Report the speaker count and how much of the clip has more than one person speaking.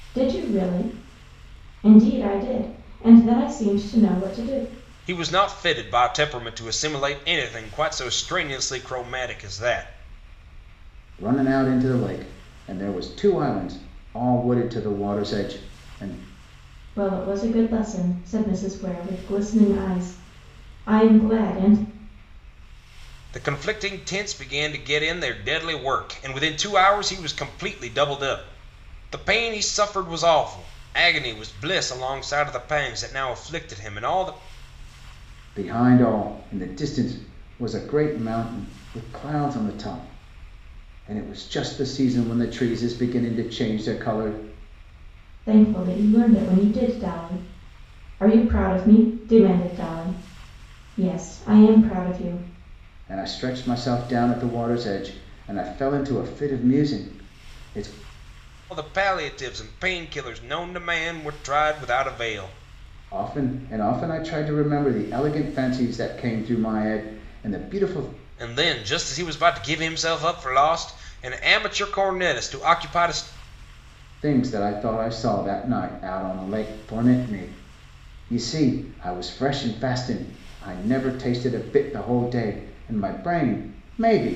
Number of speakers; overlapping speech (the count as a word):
three, no overlap